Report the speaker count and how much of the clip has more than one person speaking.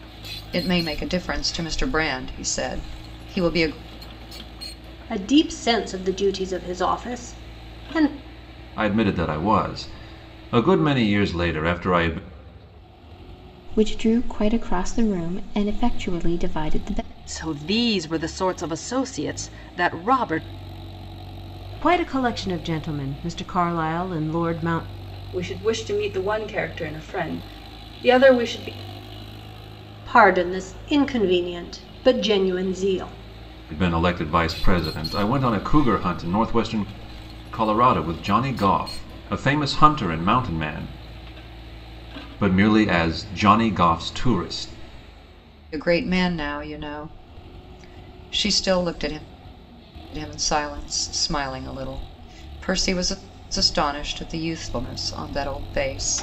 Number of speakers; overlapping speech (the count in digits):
7, no overlap